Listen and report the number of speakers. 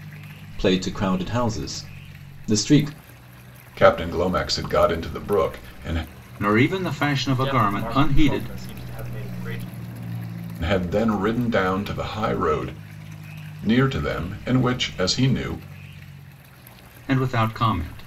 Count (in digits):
4